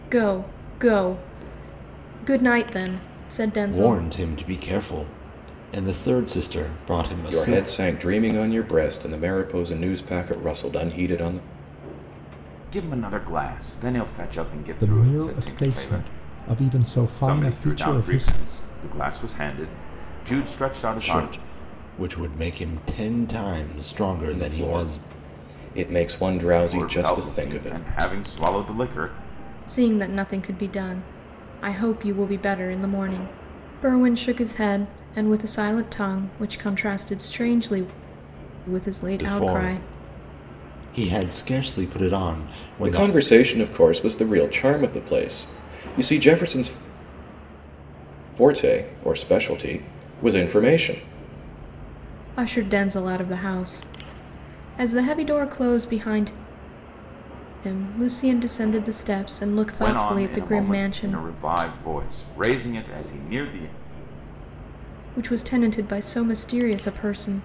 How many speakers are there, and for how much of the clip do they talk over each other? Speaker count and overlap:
5, about 12%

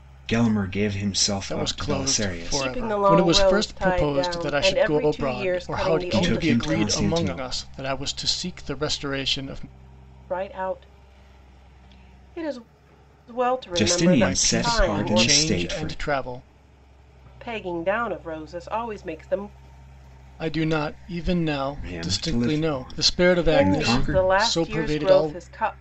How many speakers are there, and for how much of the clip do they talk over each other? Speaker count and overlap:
3, about 47%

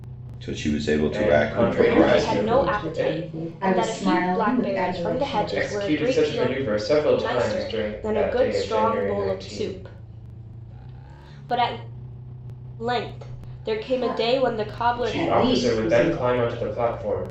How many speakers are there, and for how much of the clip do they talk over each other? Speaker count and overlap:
4, about 60%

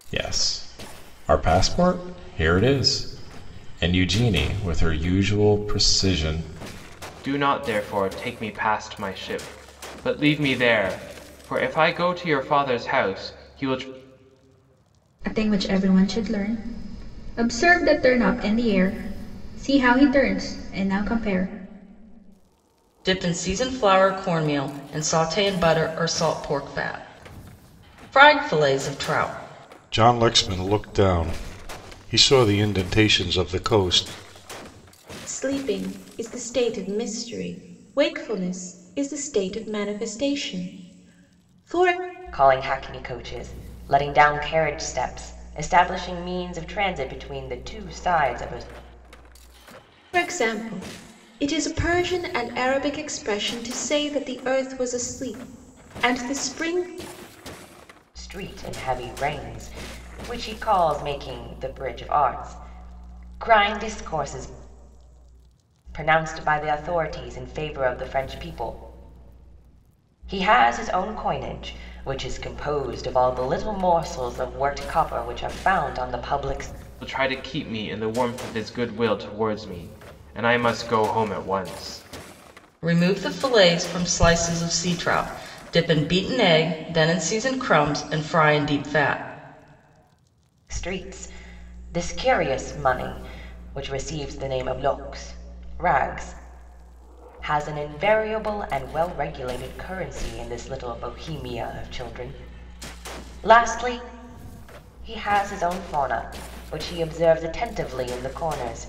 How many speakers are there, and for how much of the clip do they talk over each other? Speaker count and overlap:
7, no overlap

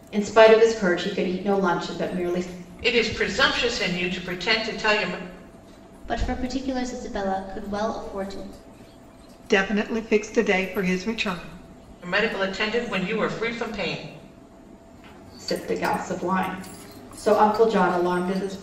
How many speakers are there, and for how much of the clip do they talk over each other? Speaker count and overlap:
4, no overlap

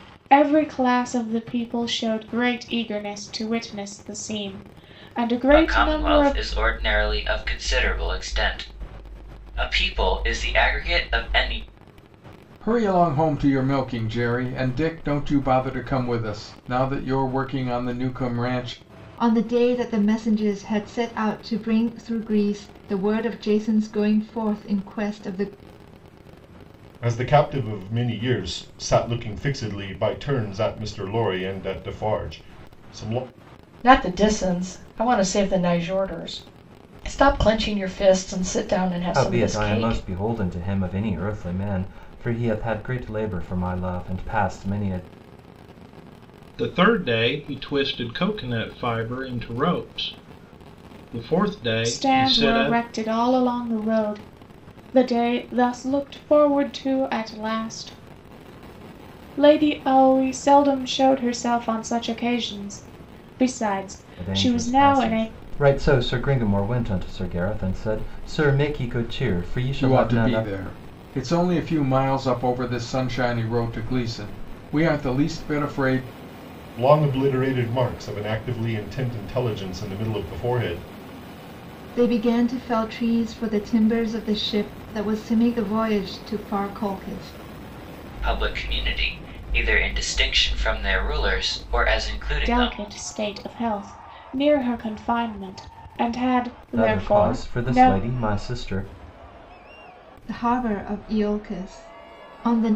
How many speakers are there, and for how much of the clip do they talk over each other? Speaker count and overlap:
8, about 6%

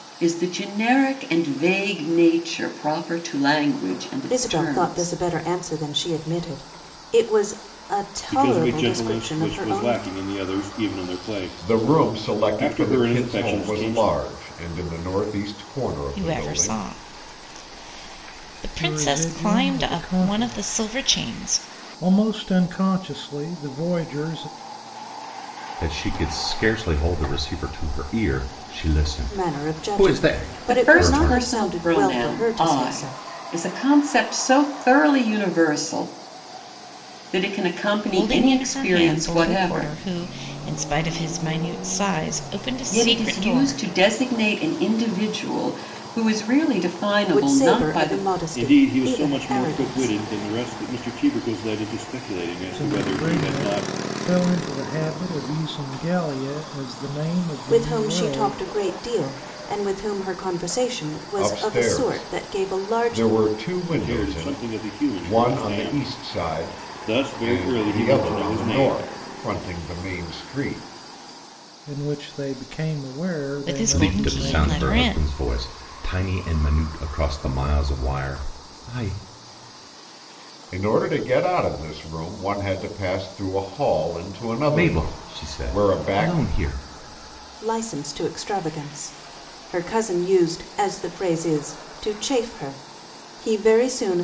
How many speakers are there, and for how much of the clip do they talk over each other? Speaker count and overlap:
7, about 32%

